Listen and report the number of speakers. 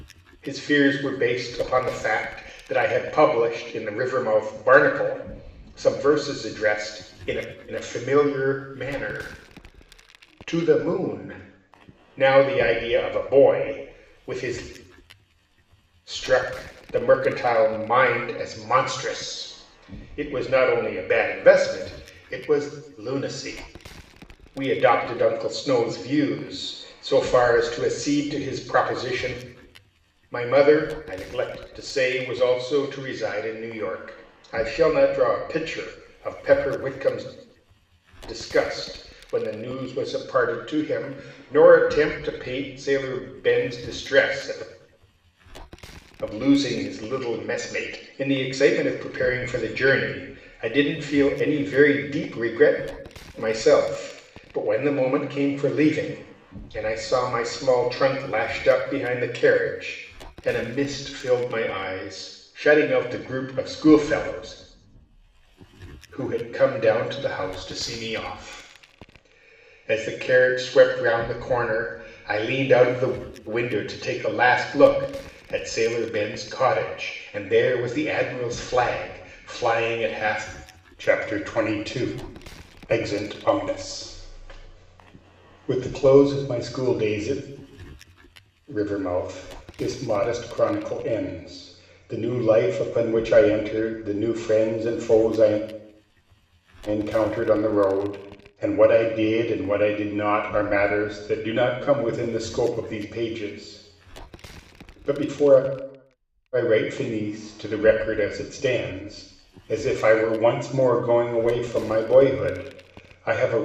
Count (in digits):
1